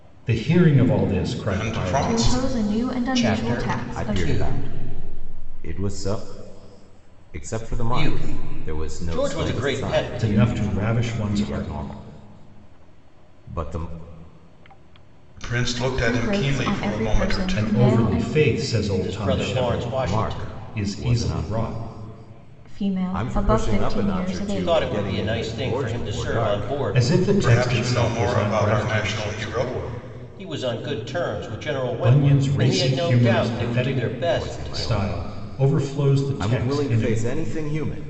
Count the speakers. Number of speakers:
5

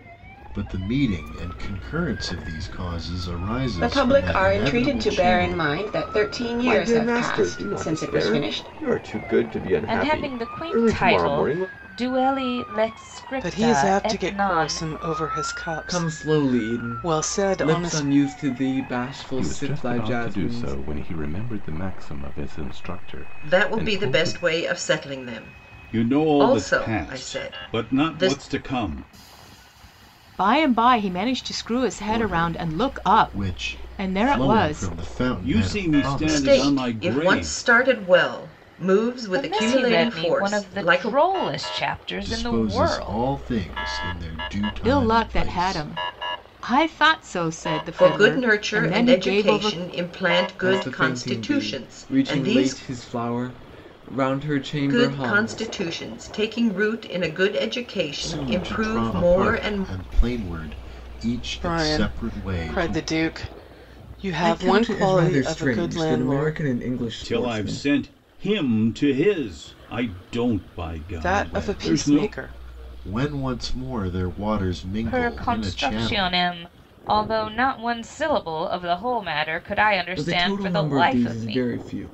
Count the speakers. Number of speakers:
10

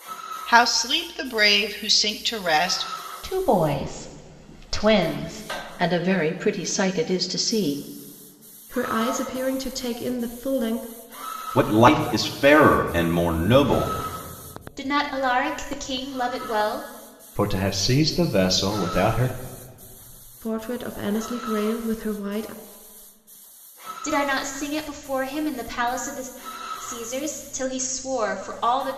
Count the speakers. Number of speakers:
7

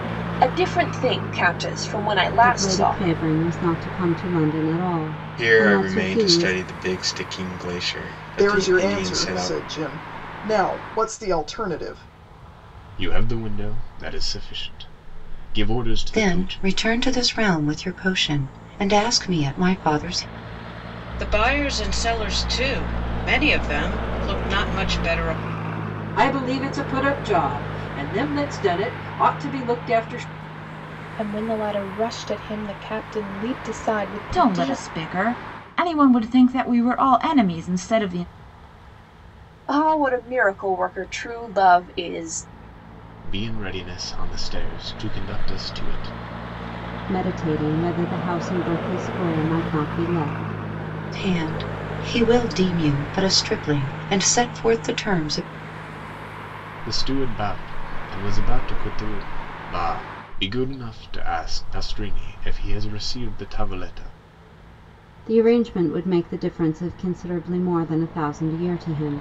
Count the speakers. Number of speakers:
10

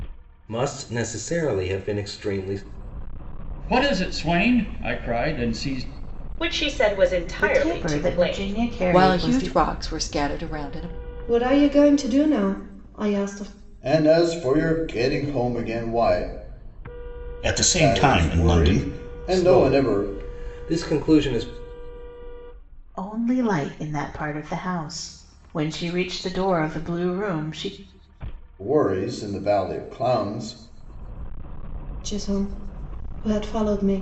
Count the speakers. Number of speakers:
8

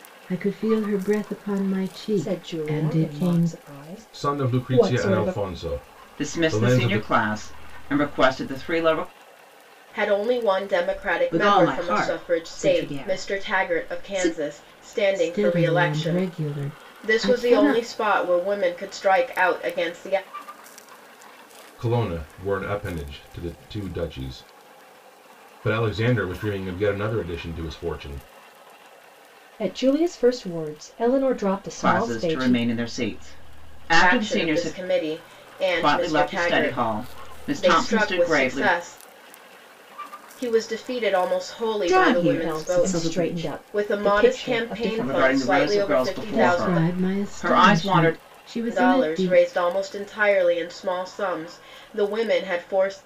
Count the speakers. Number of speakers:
6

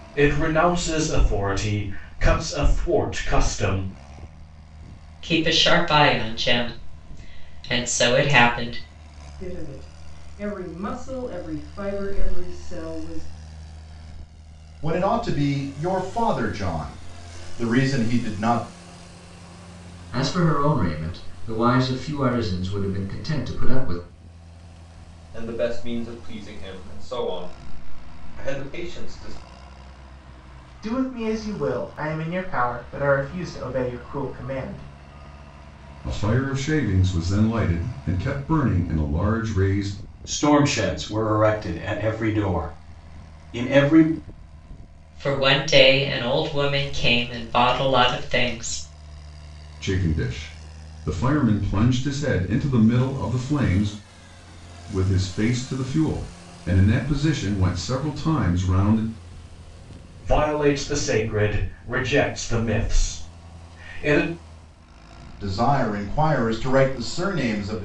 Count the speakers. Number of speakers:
9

